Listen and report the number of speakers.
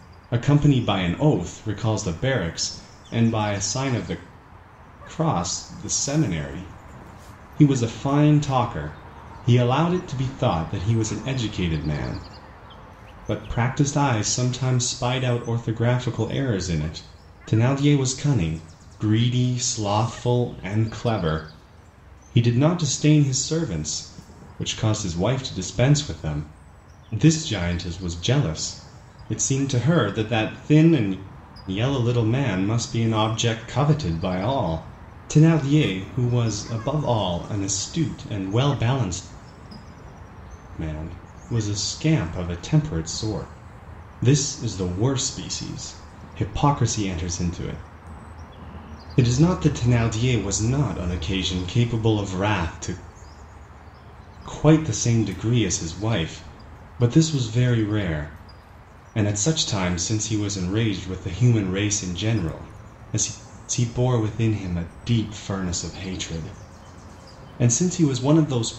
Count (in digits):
1